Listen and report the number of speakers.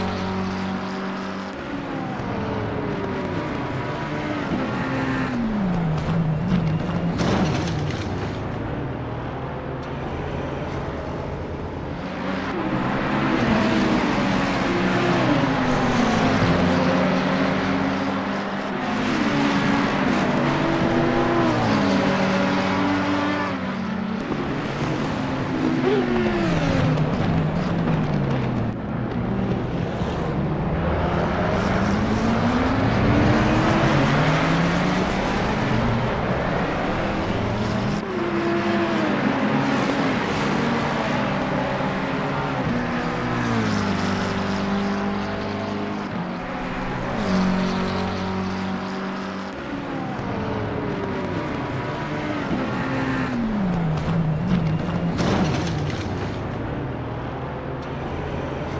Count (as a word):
zero